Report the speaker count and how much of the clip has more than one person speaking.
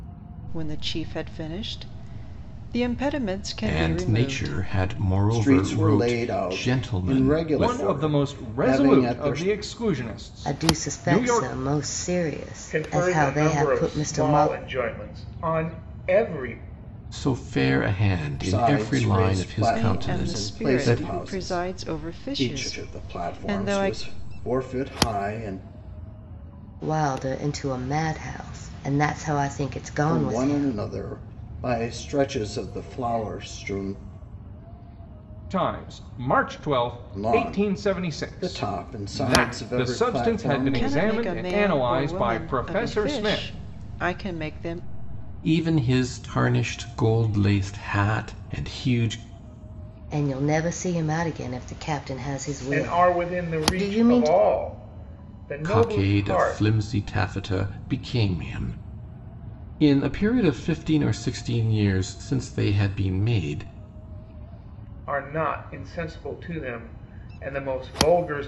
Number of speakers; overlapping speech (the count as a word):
six, about 35%